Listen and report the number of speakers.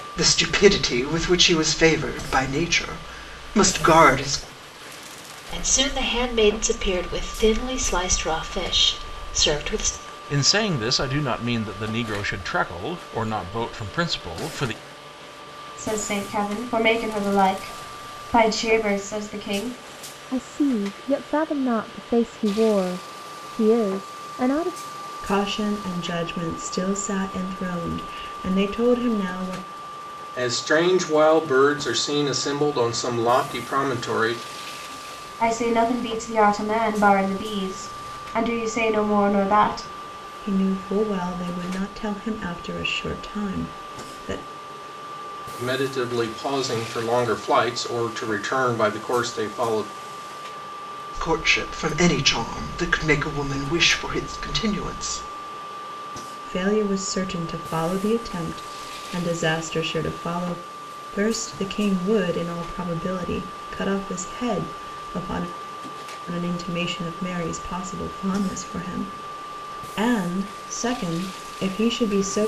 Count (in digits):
7